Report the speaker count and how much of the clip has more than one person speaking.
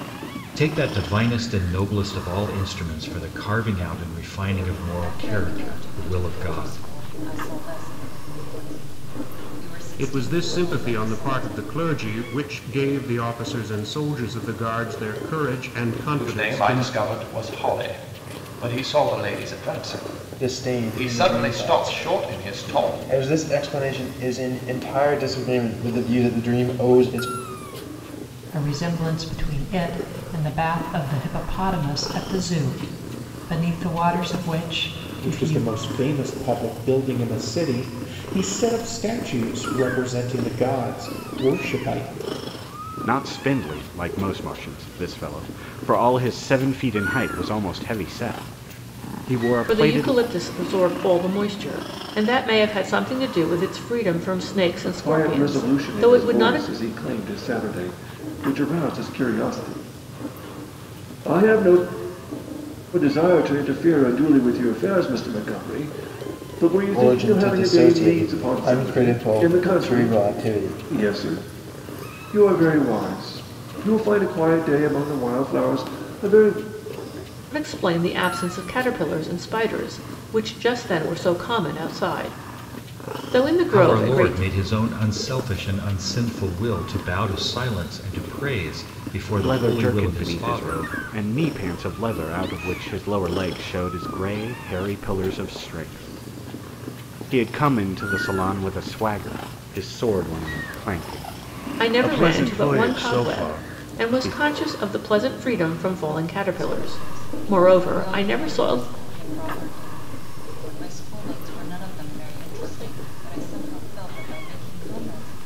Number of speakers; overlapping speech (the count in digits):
10, about 18%